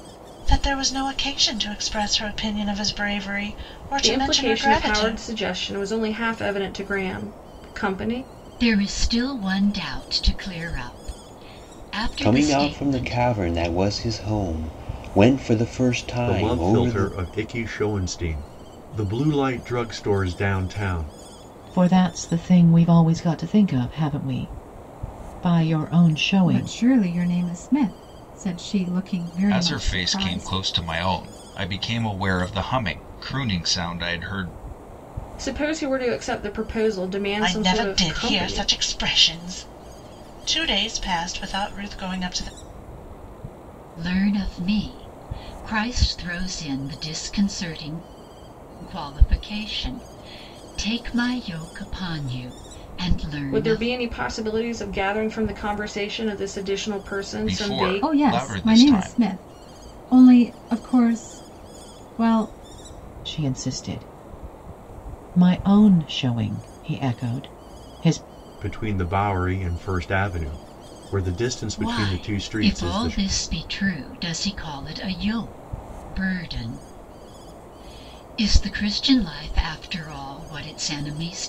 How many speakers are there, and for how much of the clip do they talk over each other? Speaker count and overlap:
8, about 12%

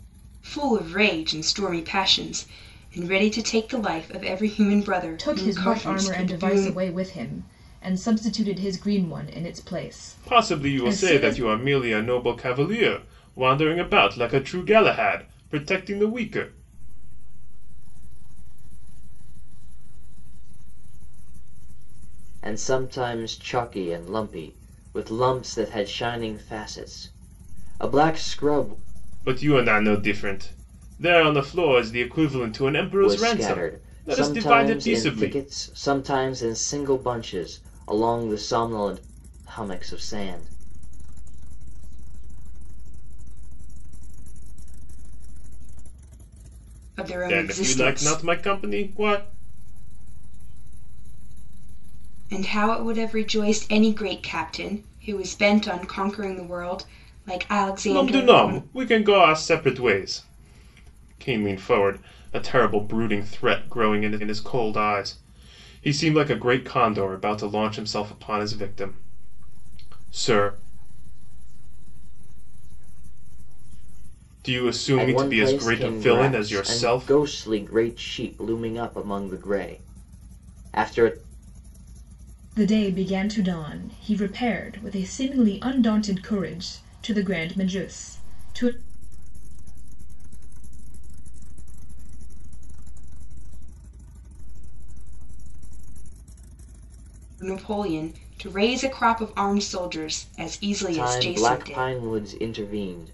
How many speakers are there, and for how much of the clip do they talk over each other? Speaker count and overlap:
5, about 22%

